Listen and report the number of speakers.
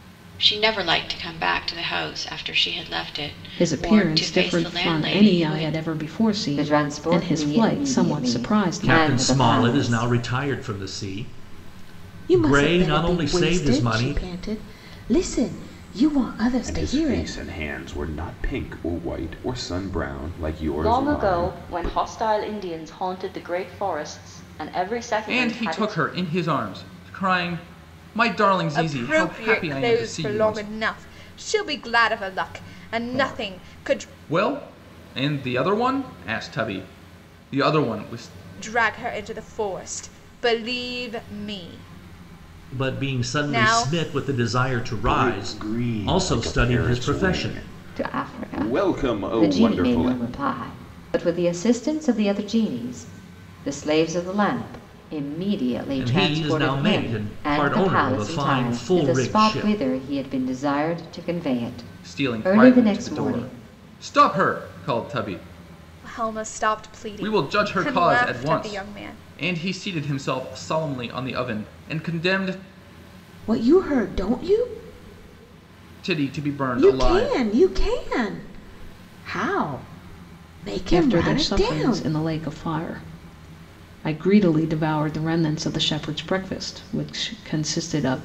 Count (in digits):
9